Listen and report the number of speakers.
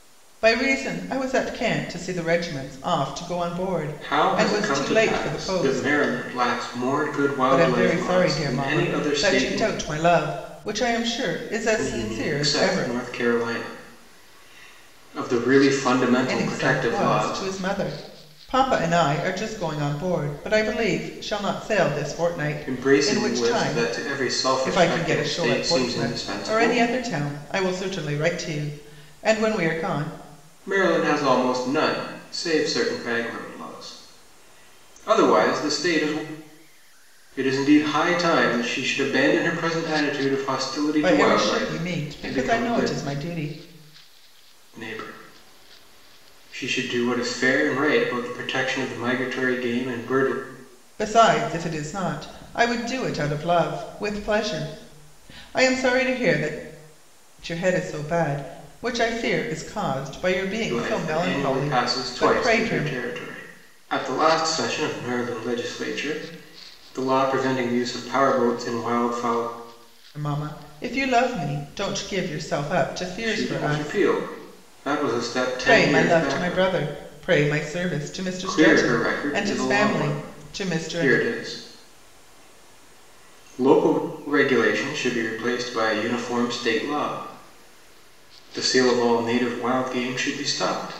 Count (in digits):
2